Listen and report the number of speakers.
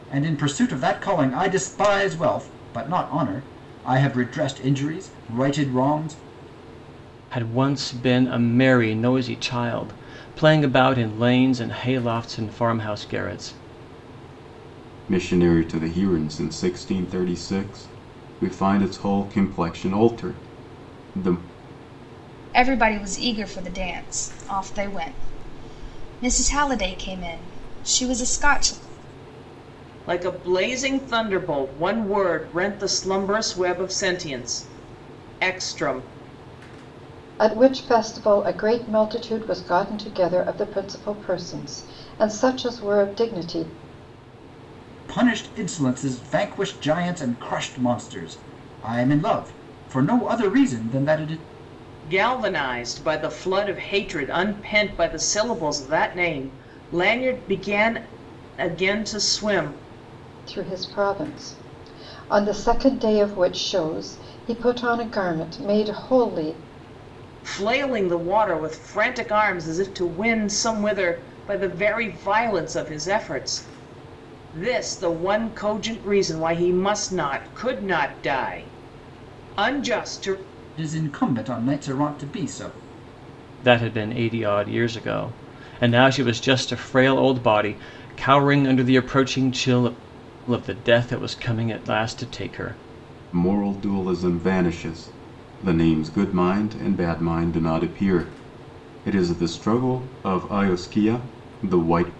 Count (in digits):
6